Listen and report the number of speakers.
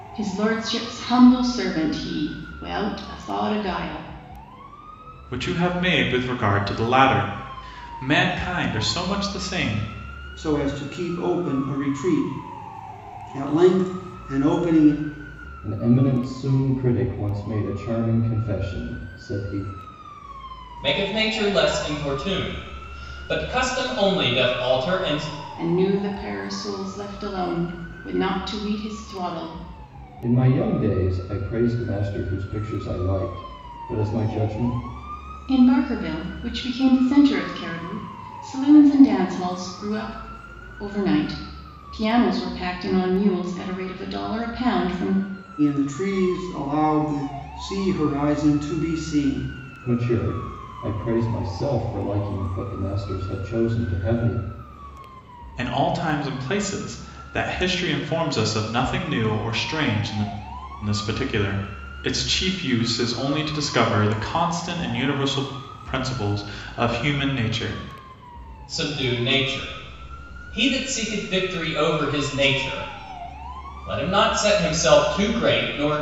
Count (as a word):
five